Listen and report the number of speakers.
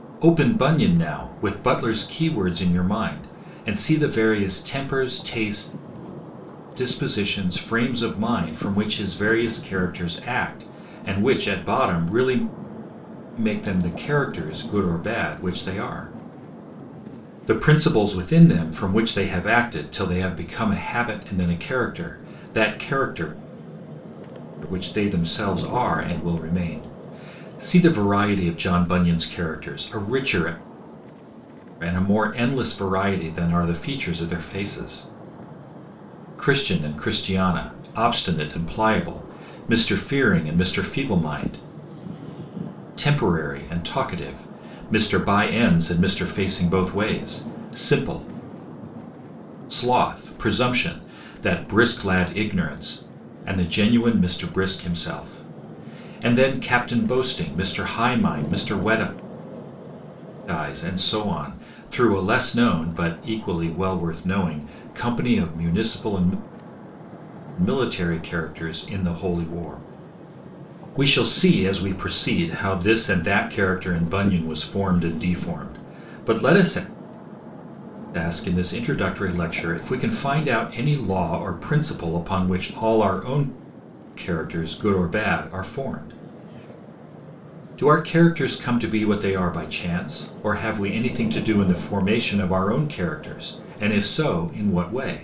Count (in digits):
1